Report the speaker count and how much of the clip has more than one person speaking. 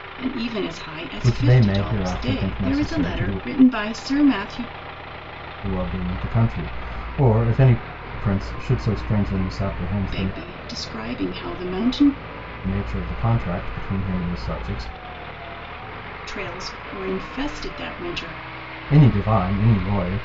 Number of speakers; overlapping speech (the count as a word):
two, about 13%